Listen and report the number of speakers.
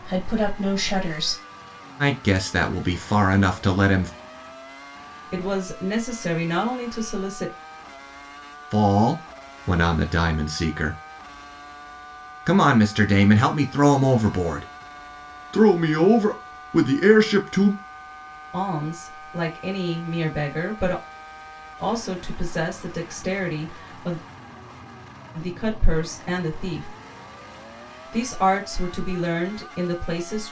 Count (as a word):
three